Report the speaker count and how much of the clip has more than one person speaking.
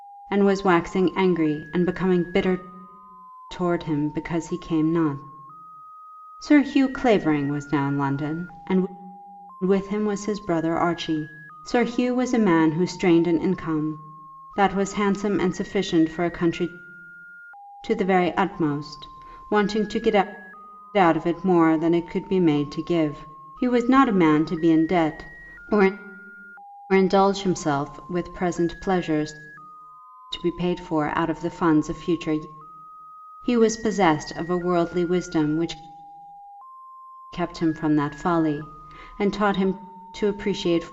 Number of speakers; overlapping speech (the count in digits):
1, no overlap